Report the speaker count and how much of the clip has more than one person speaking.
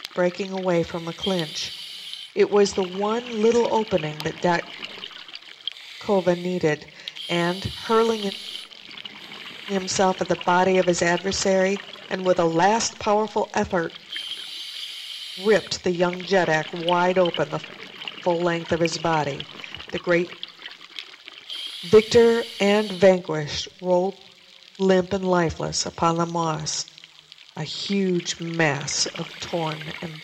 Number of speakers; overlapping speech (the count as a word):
one, no overlap